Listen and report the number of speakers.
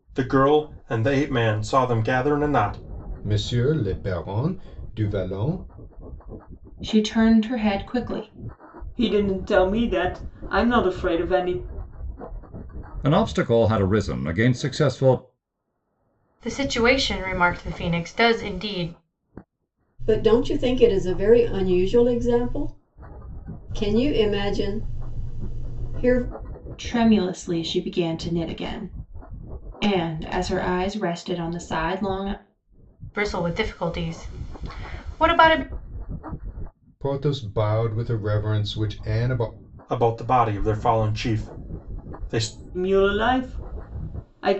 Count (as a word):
seven